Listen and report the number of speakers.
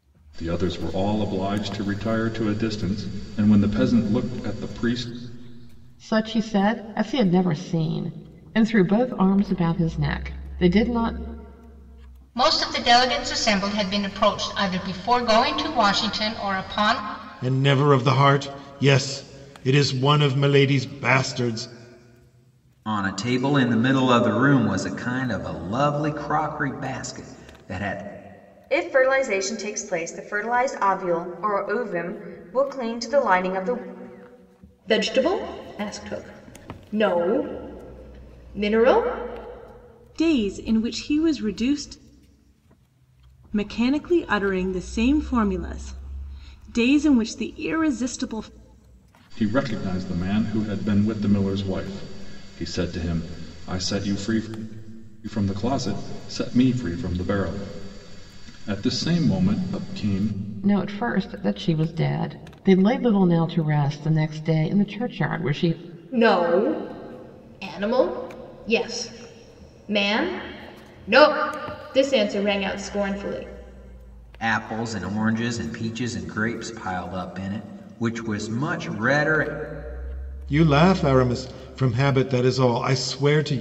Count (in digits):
8